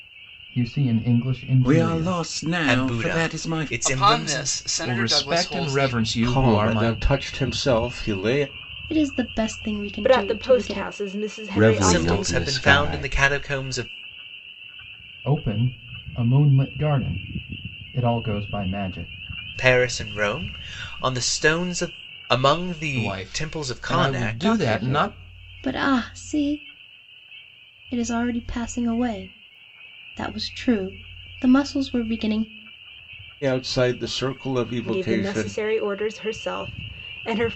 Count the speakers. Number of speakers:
9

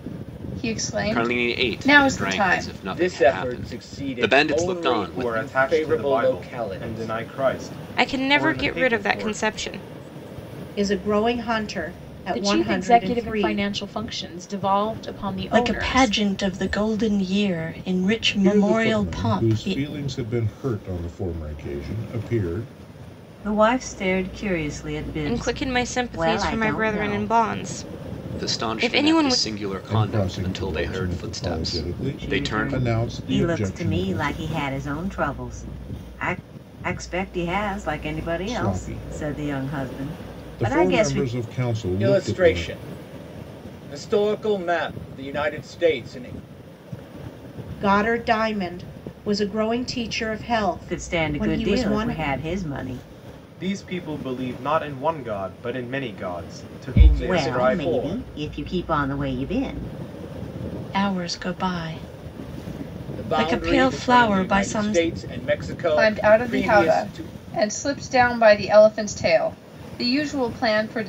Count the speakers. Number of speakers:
10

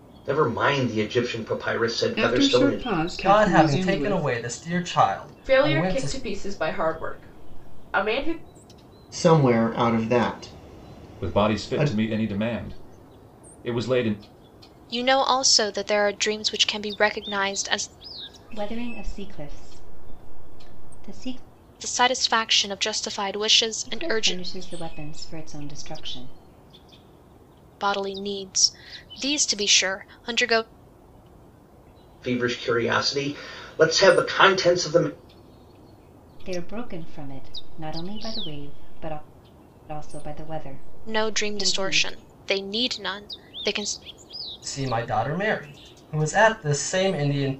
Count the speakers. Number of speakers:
8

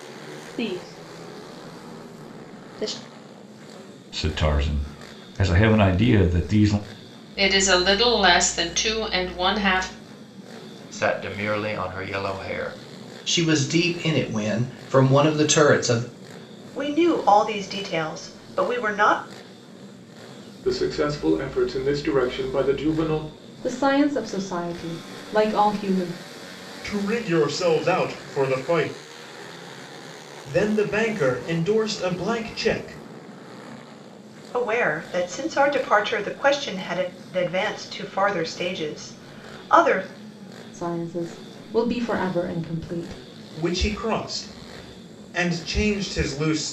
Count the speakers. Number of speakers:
9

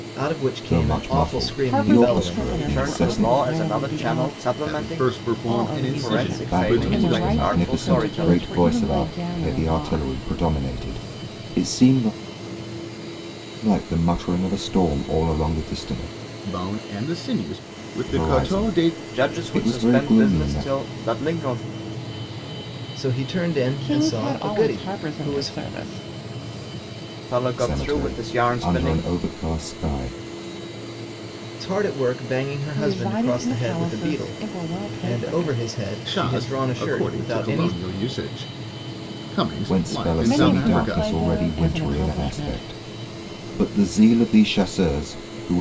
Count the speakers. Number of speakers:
5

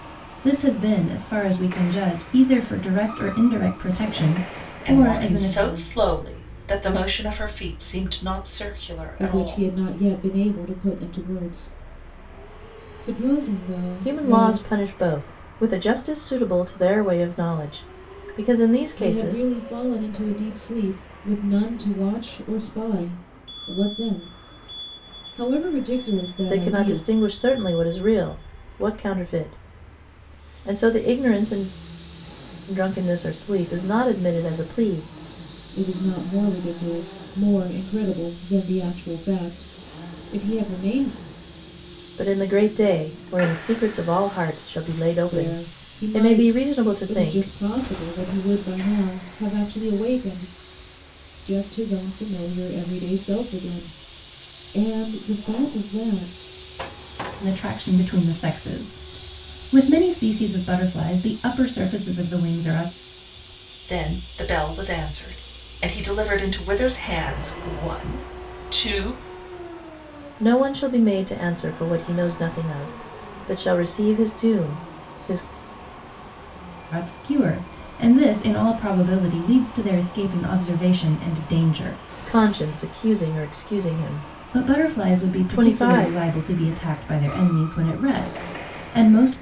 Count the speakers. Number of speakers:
4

